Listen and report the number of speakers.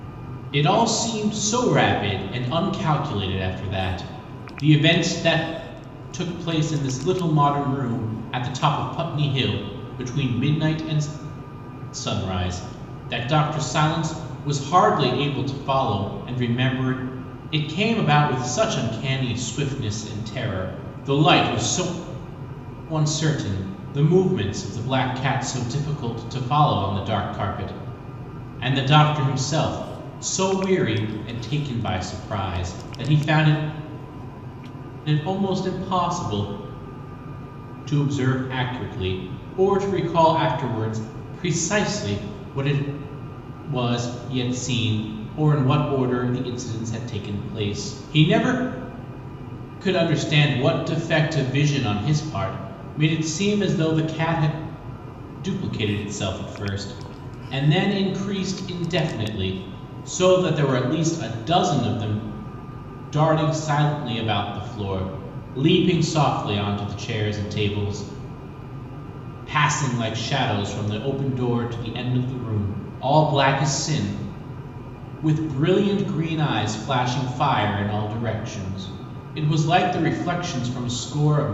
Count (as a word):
one